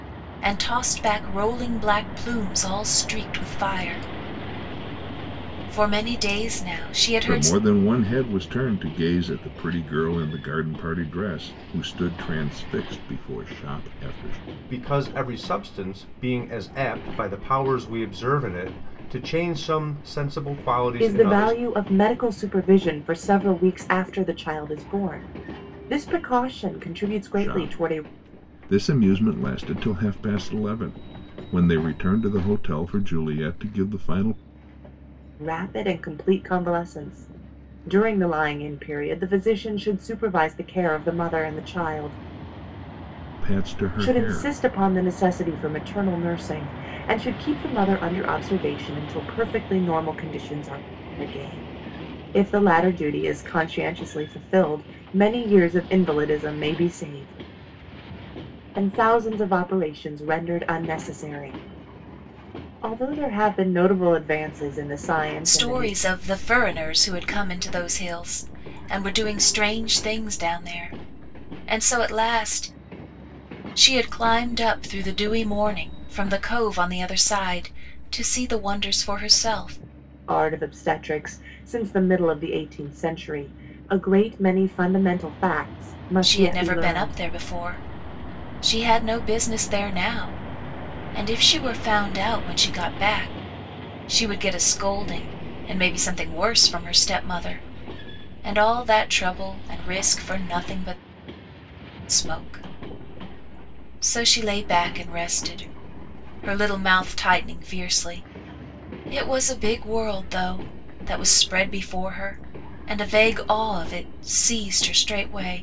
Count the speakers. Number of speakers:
4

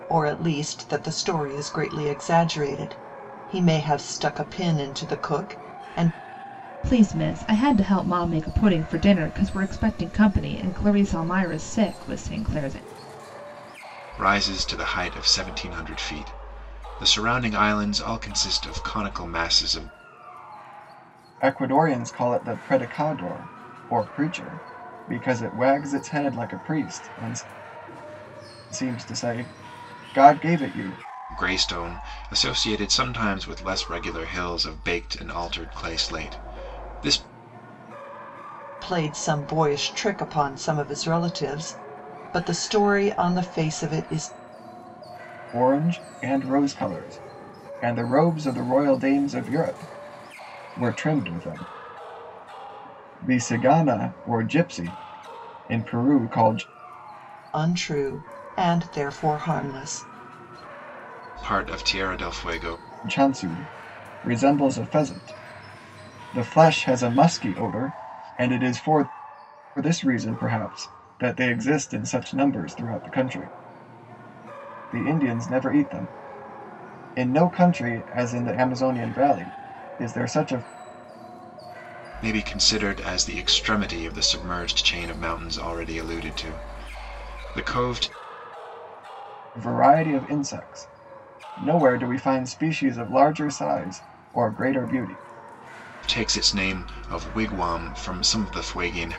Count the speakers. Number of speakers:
4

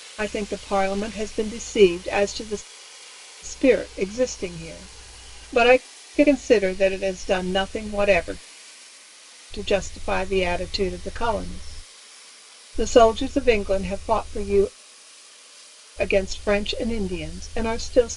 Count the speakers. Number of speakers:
1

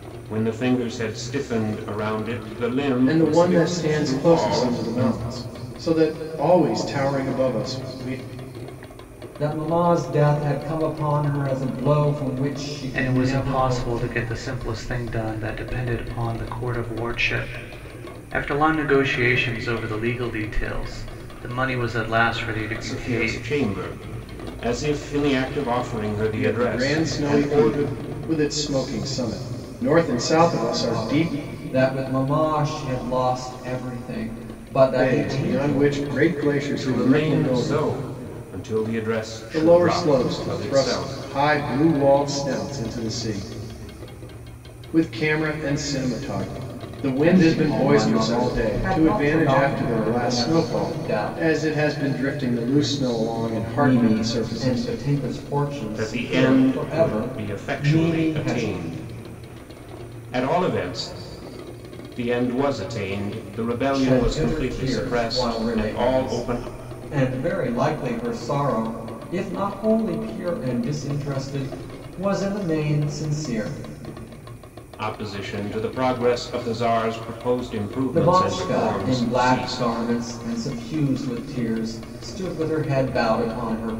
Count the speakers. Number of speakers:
4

